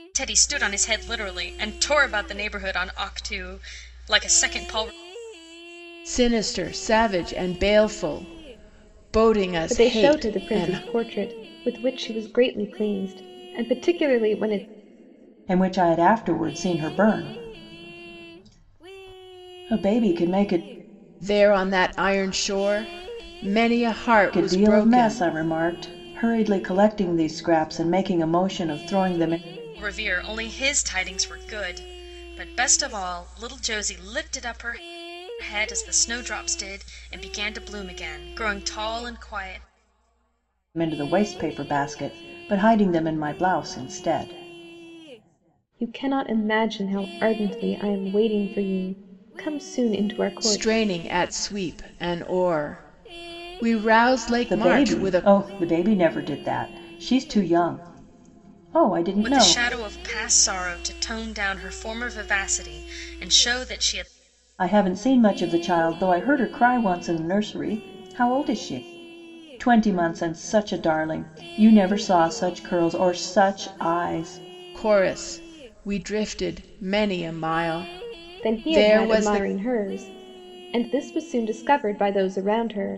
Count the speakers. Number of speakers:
4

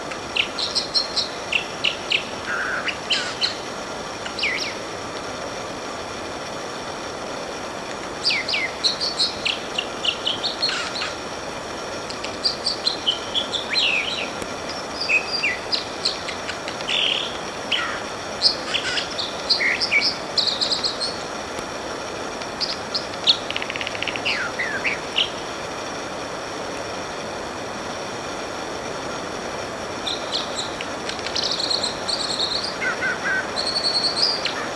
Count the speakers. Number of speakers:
0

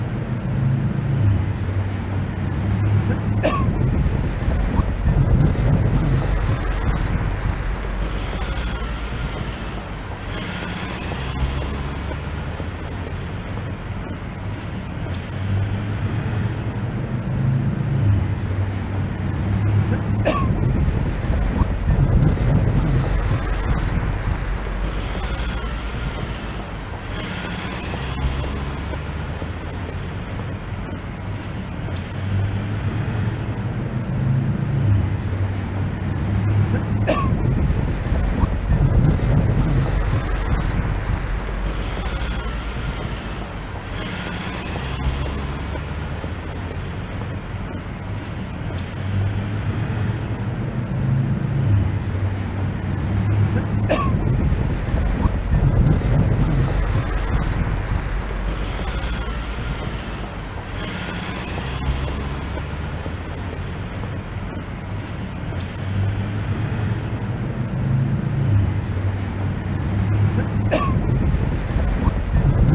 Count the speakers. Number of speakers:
0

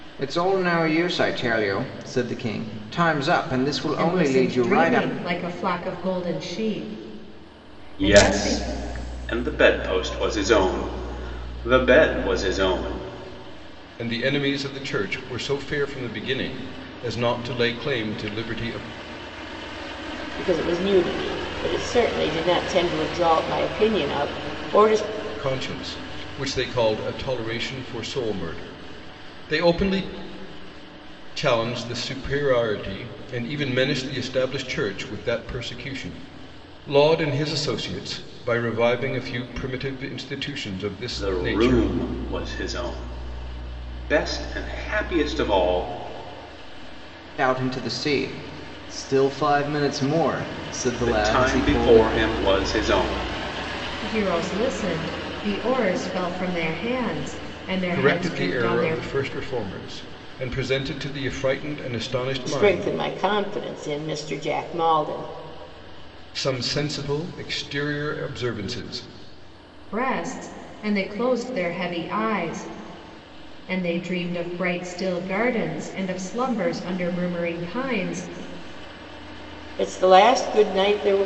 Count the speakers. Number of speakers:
5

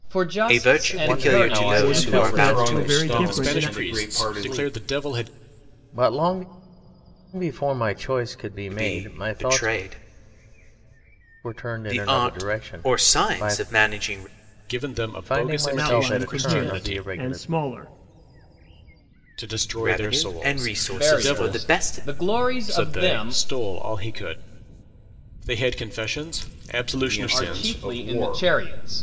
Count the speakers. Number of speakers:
6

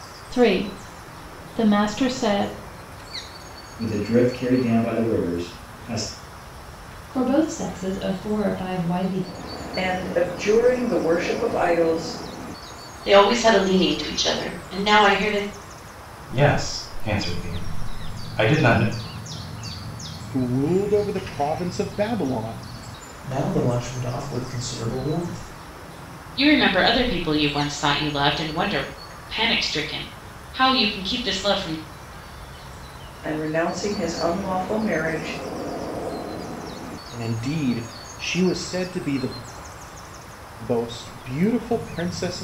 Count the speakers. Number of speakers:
9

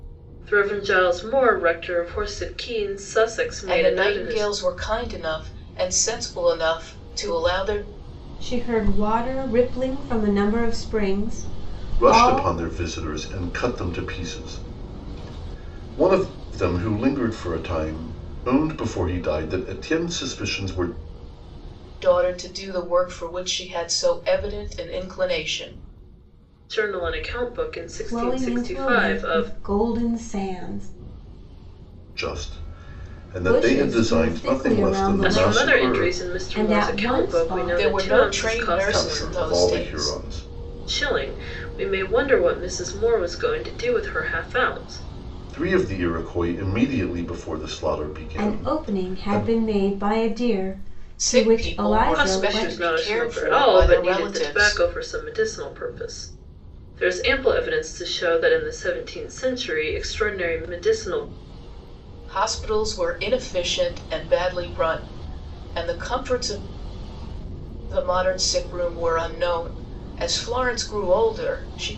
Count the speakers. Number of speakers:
4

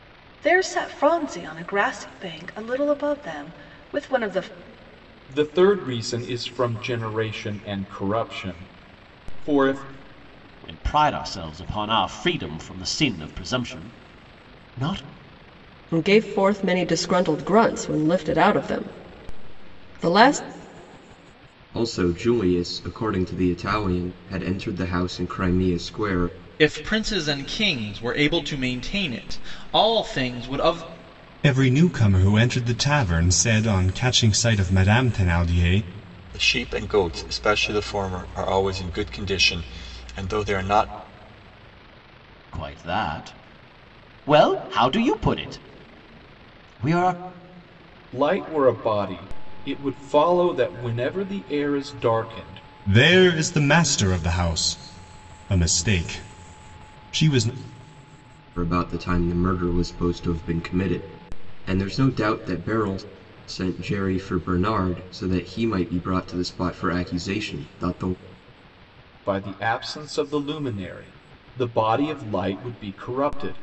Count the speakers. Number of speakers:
8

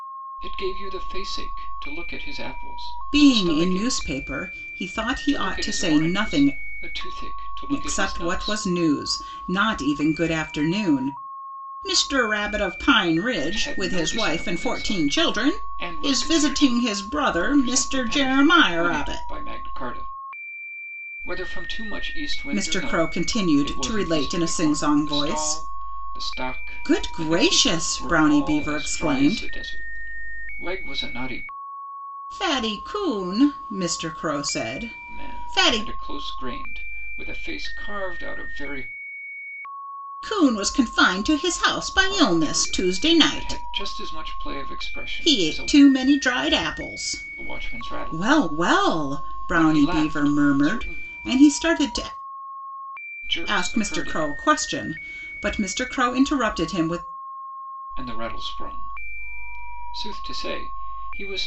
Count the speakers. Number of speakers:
2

